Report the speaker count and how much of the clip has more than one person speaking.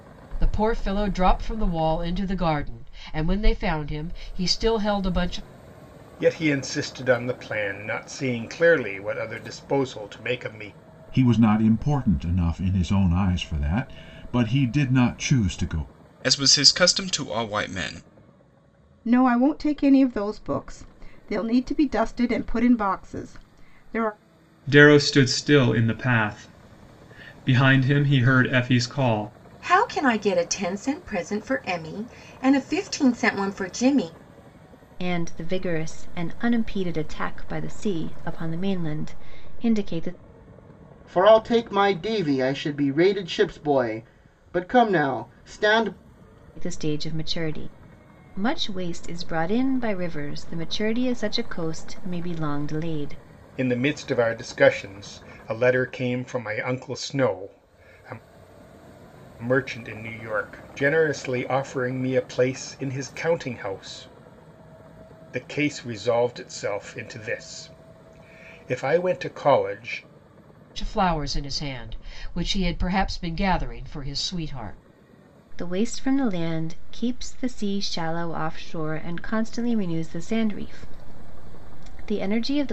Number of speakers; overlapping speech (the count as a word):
nine, no overlap